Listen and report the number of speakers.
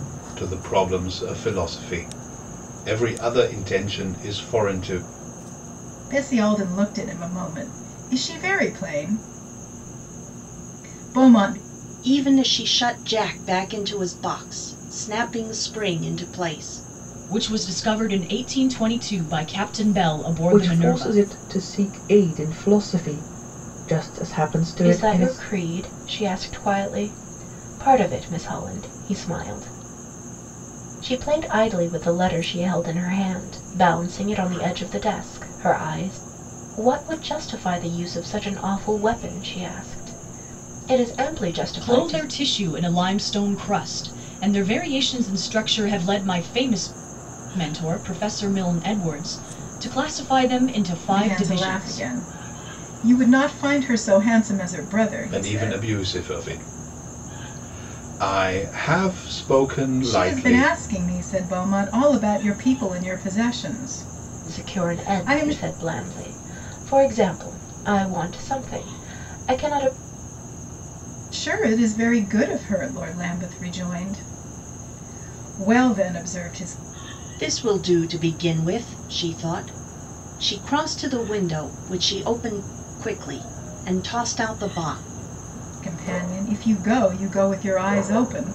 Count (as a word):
six